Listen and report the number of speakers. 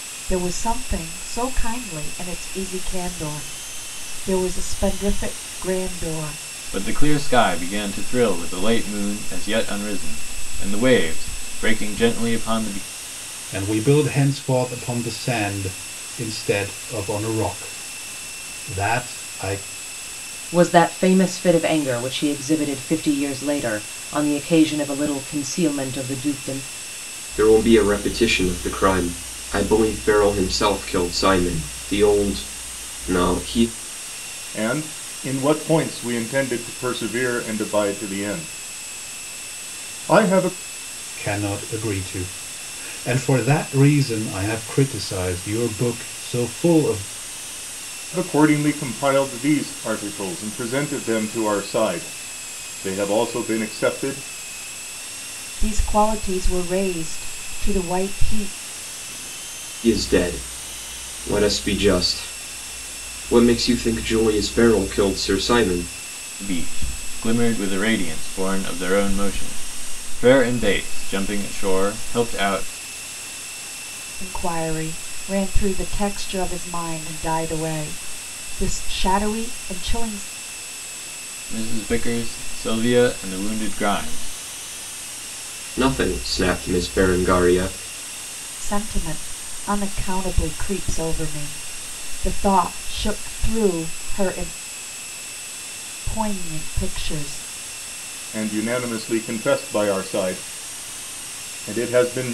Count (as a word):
six